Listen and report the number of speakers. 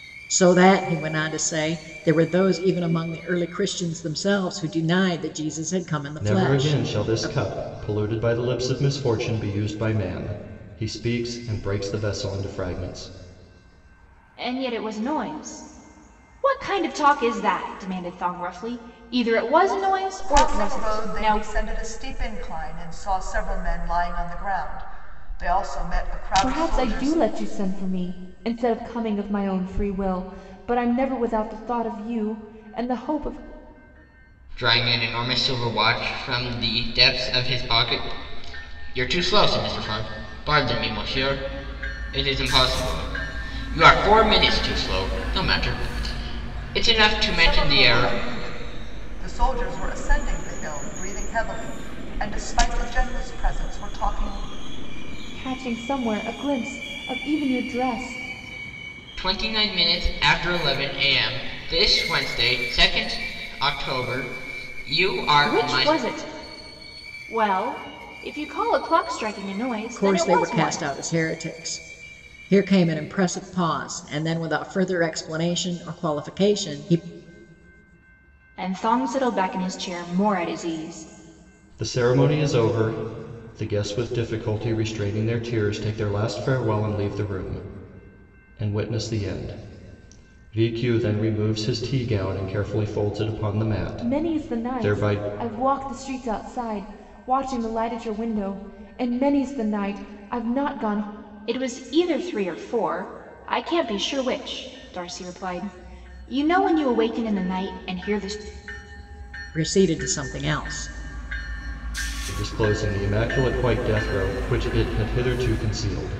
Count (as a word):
six